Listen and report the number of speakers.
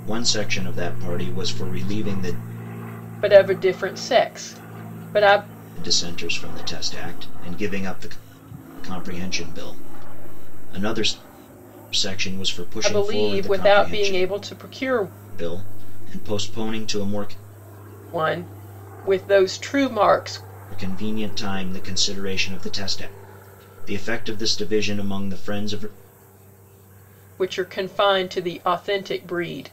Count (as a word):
two